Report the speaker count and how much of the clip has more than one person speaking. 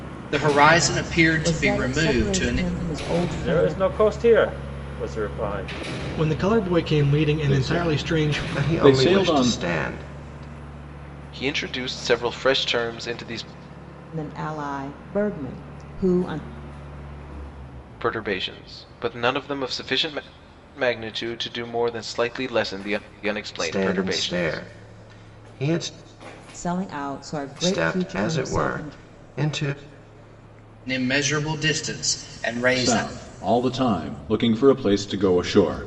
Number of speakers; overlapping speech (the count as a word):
seven, about 18%